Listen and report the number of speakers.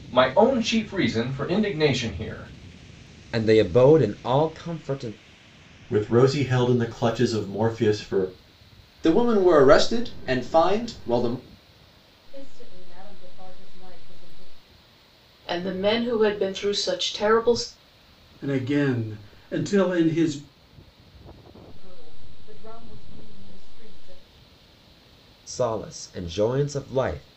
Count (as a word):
seven